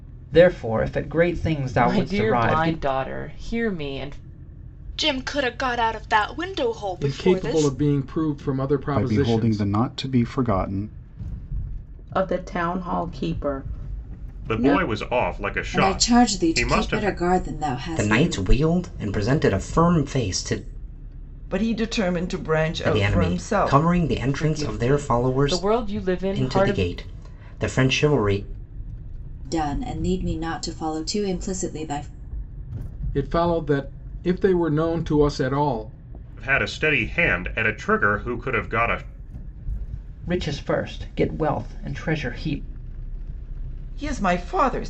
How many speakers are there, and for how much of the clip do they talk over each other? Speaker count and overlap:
10, about 18%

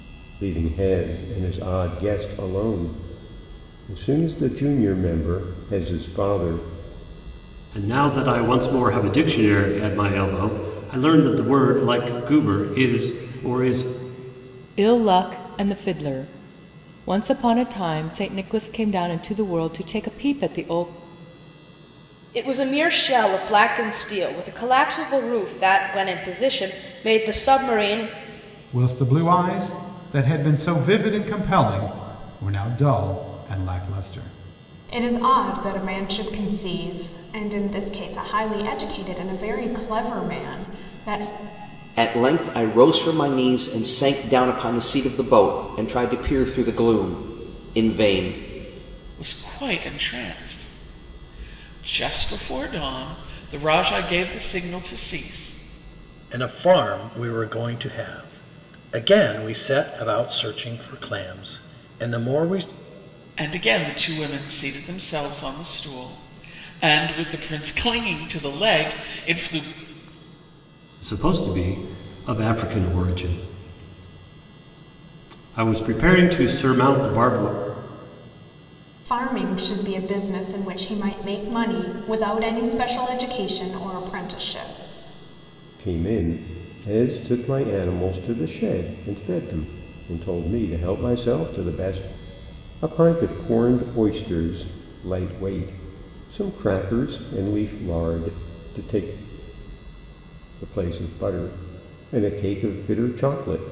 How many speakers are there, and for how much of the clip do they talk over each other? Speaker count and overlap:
9, no overlap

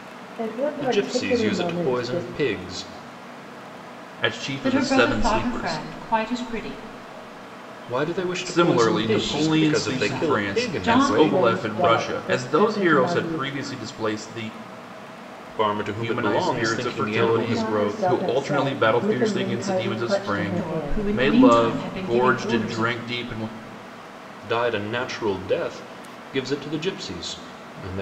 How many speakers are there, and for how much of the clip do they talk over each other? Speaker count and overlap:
4, about 53%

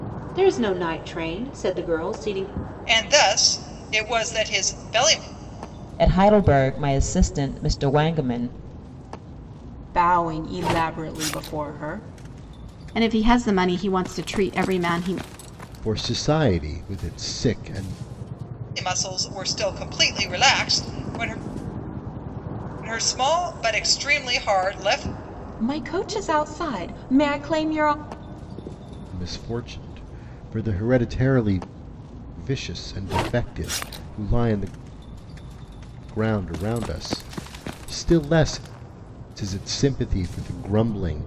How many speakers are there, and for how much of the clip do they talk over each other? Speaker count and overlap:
6, no overlap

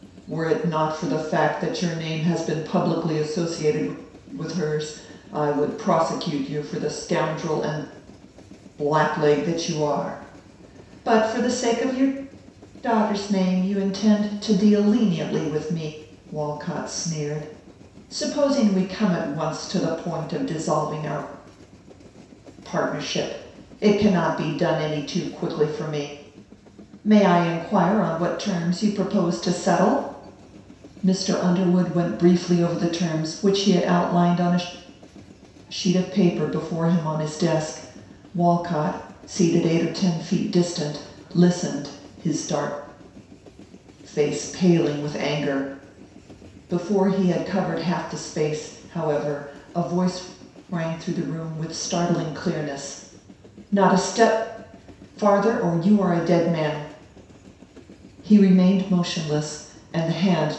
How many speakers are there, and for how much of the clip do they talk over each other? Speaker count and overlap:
1, no overlap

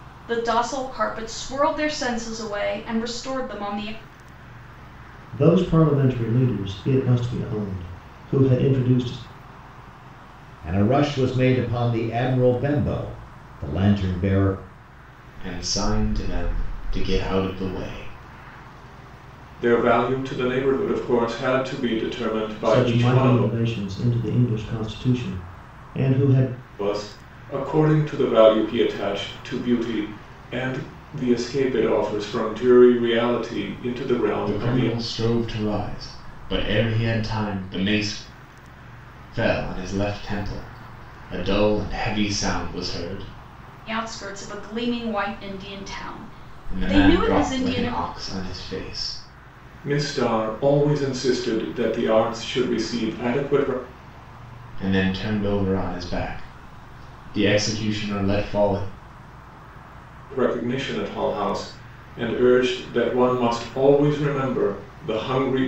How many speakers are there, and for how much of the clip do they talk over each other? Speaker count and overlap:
5, about 4%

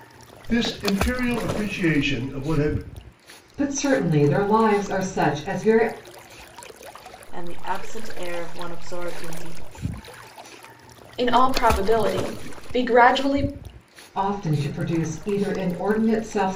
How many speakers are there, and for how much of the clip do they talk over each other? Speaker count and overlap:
4, no overlap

